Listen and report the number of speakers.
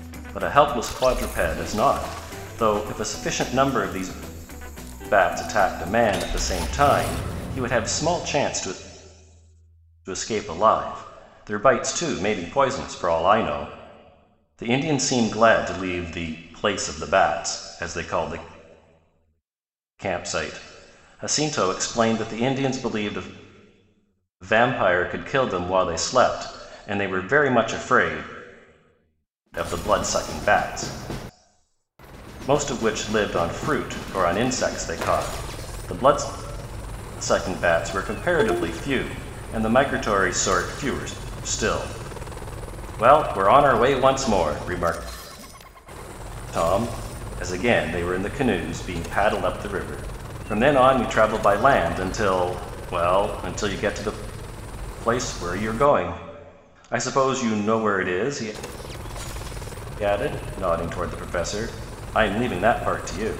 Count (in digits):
1